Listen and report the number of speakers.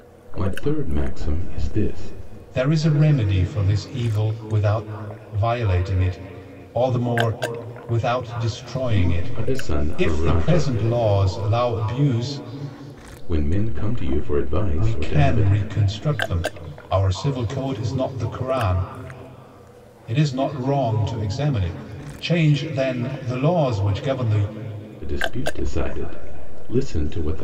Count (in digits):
2